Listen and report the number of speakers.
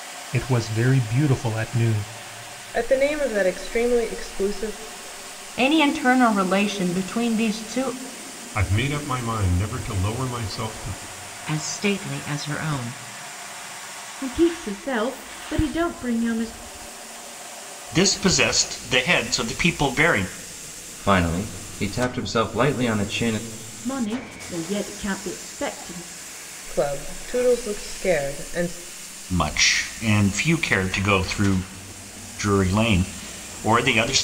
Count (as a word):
eight